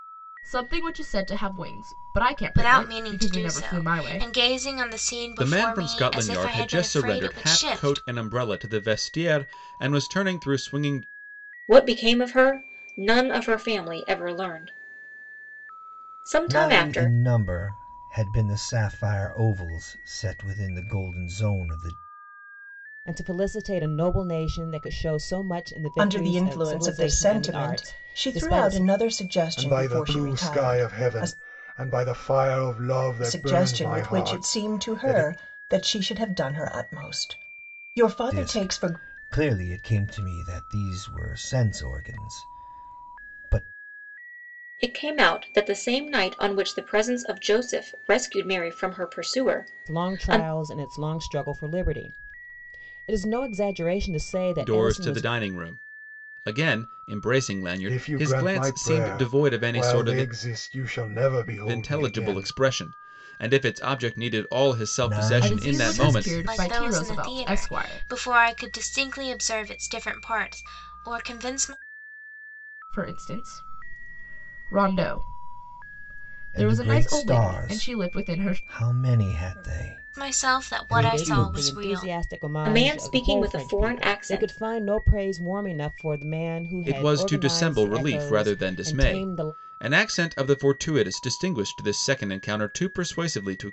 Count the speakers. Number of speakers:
8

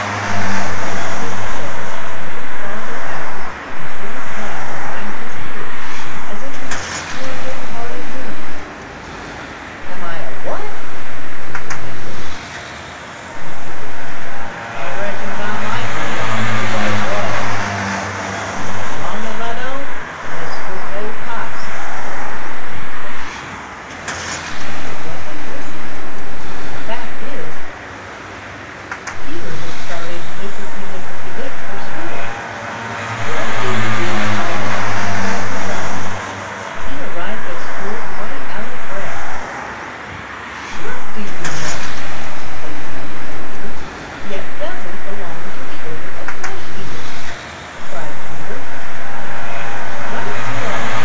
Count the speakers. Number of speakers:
1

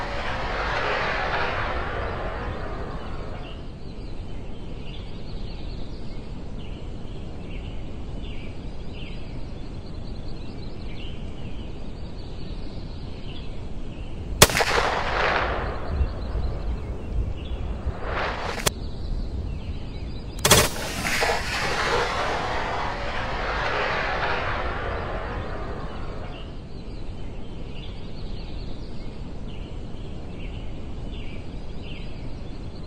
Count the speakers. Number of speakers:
0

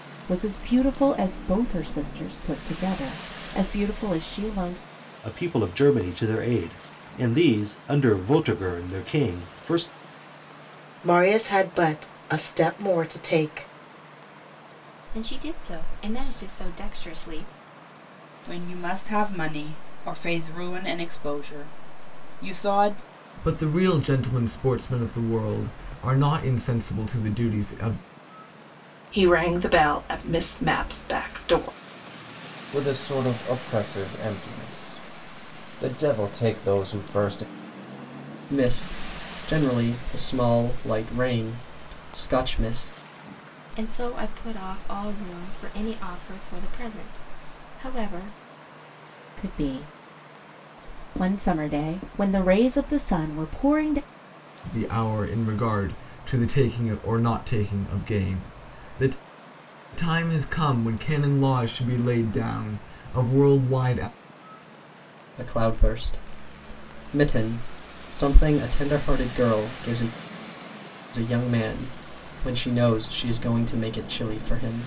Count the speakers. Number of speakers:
9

